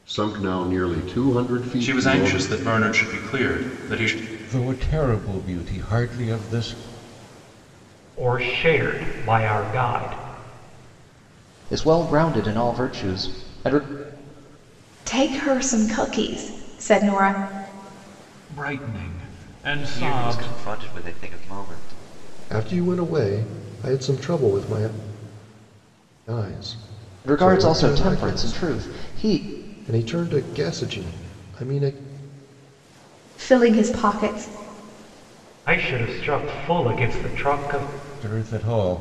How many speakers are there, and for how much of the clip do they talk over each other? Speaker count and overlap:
9, about 8%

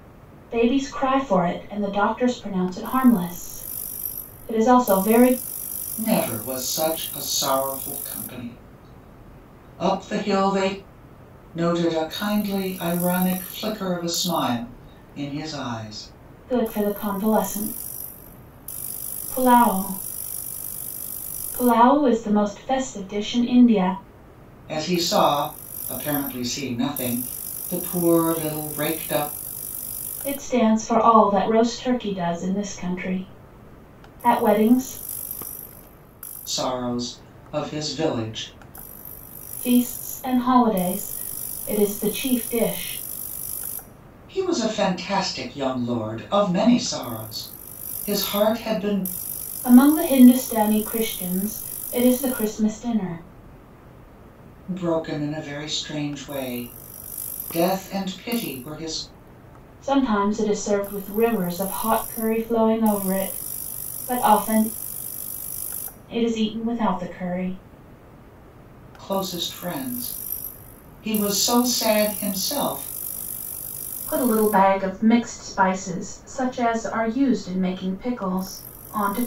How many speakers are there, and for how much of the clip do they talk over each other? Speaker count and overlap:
2, no overlap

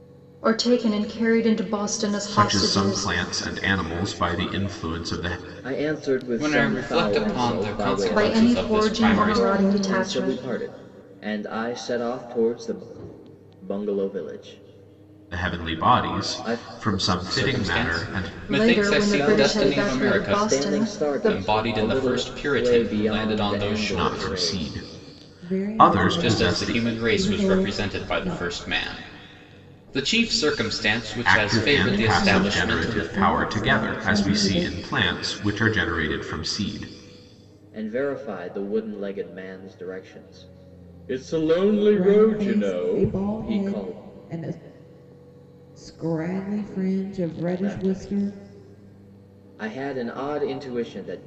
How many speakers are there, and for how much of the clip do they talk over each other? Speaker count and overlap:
5, about 44%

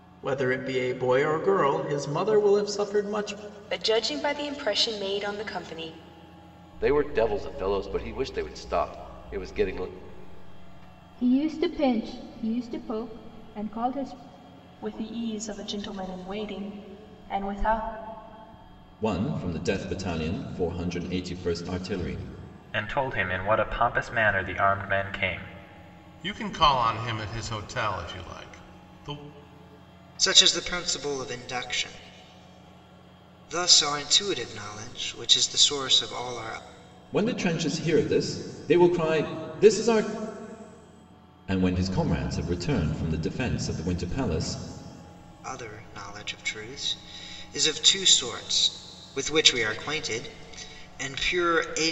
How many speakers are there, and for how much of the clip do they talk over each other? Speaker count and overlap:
9, no overlap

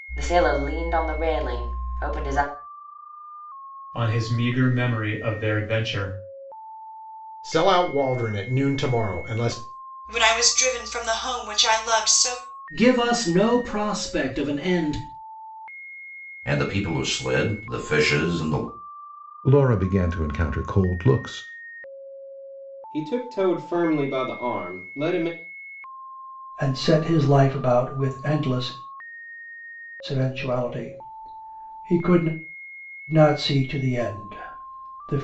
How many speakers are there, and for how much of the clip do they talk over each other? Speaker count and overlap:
9, no overlap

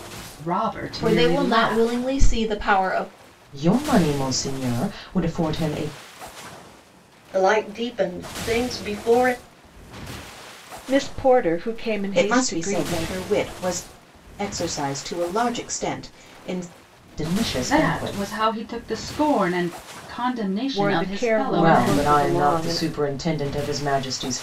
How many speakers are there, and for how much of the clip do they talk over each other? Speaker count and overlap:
6, about 20%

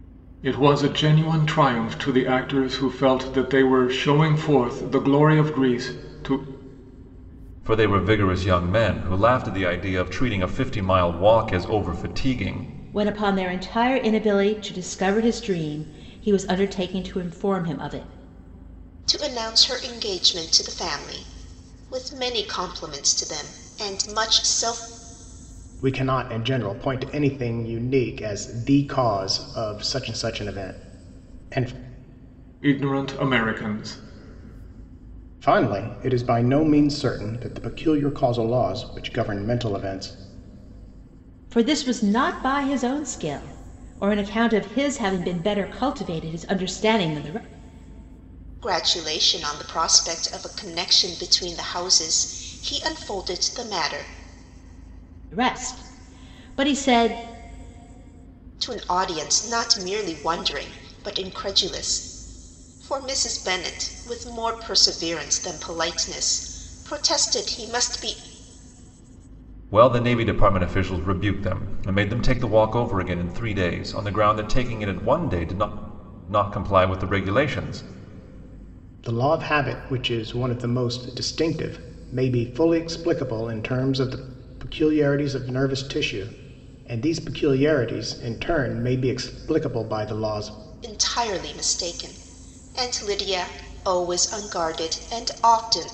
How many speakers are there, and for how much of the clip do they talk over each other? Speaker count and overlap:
5, no overlap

